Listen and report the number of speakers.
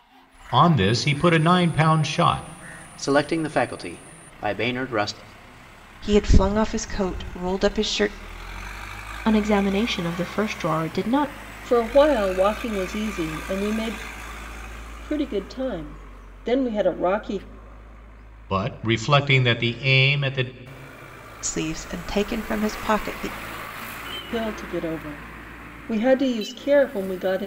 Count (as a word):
five